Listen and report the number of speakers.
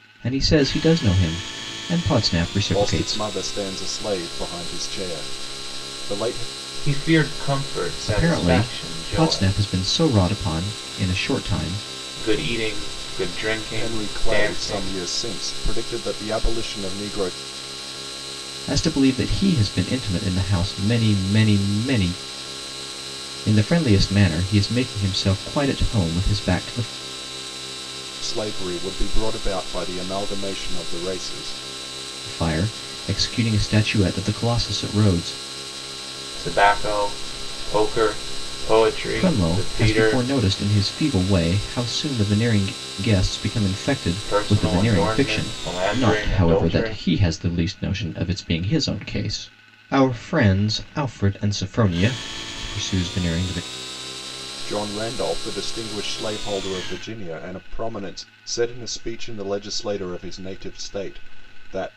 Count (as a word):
three